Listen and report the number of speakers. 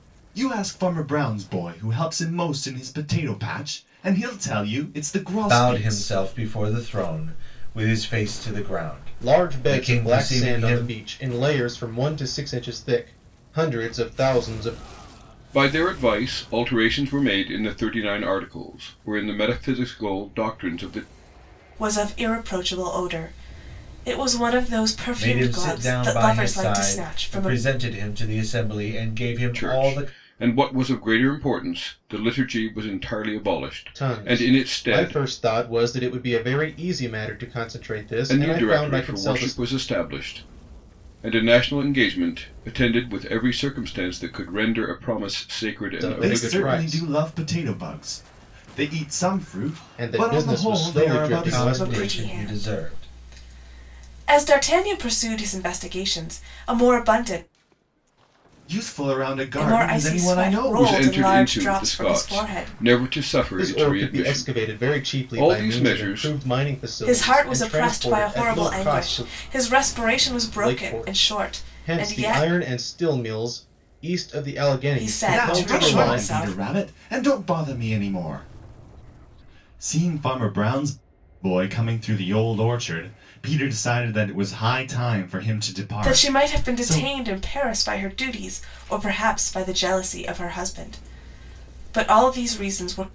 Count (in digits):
5